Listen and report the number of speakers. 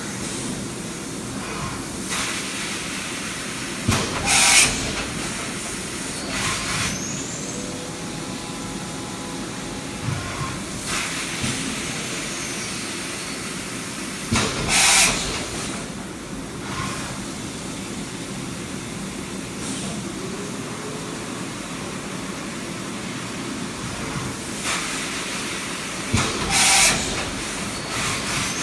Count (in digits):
0